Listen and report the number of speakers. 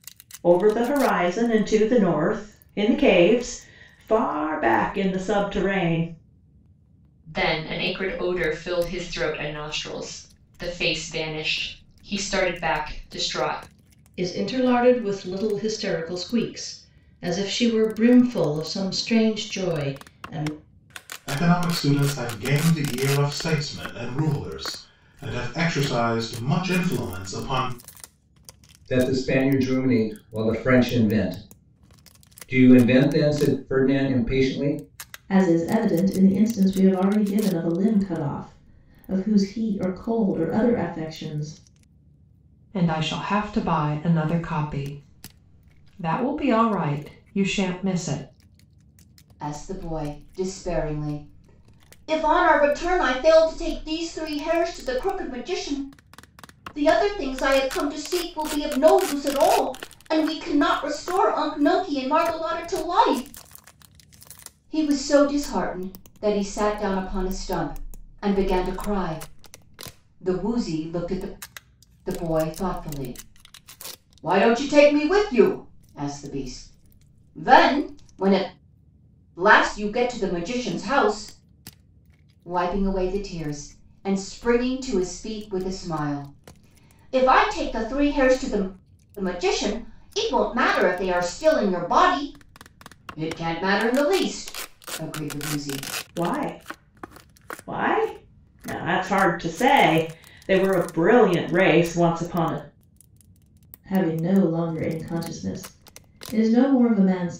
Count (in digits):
8